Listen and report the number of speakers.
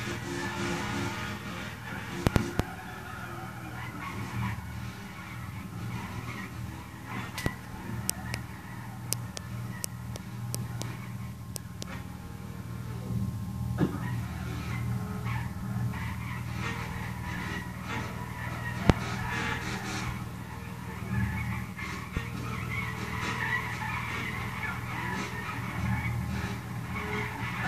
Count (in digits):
0